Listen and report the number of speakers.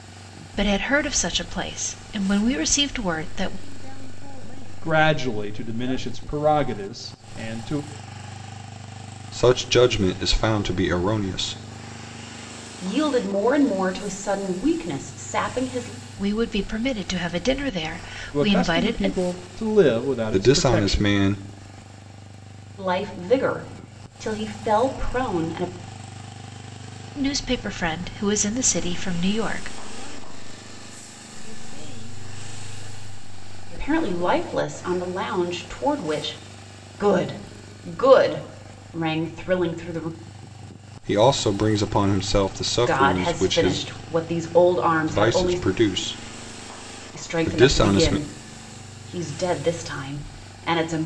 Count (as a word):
five